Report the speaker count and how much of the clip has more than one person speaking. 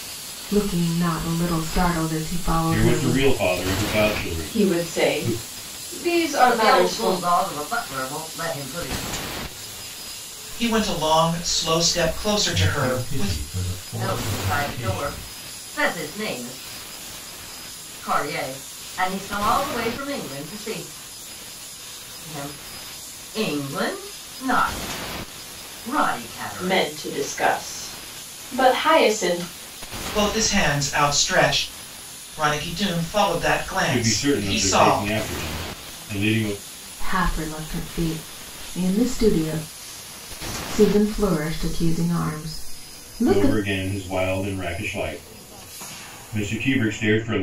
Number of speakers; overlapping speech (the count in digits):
6, about 14%